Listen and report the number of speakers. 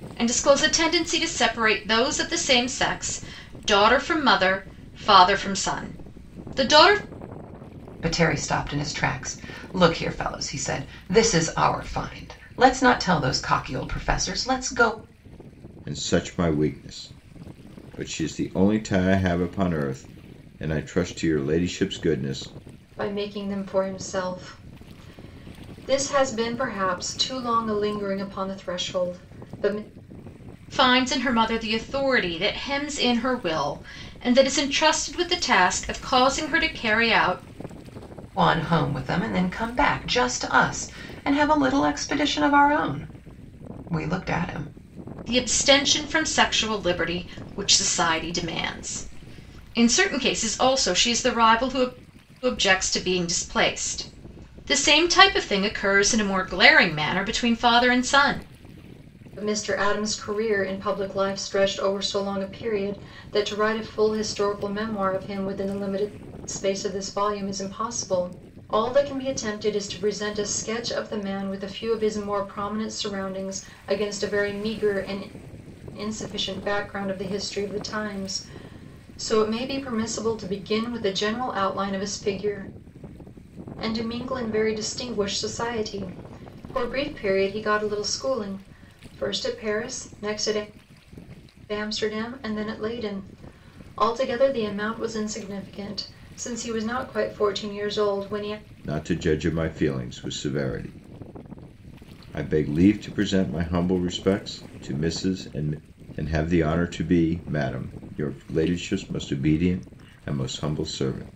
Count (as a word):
four